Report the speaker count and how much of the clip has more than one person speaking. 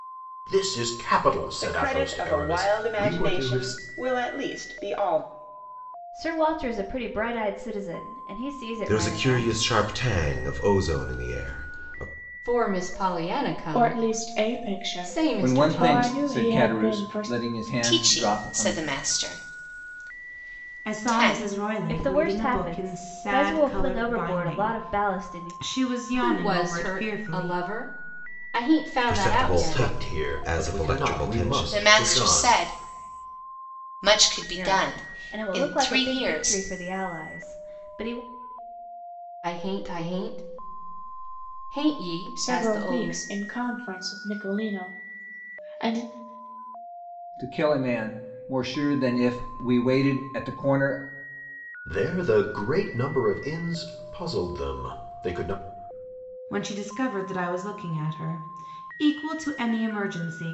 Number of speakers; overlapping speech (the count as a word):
nine, about 33%